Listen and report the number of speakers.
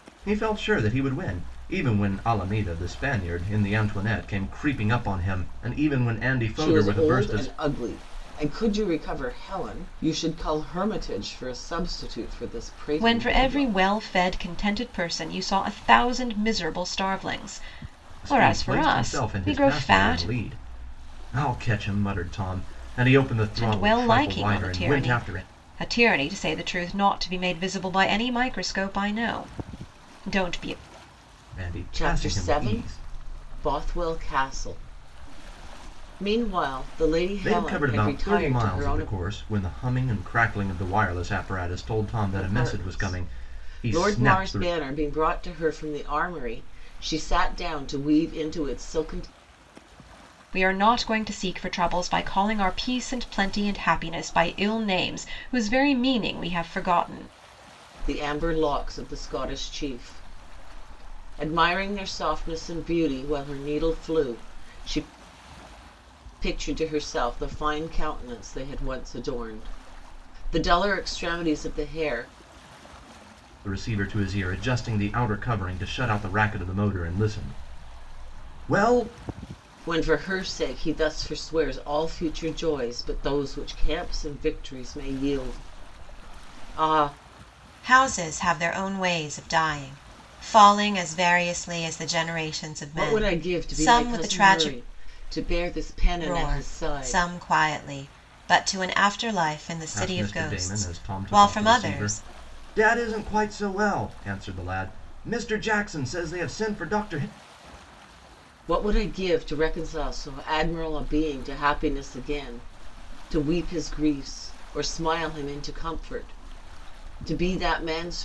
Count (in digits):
3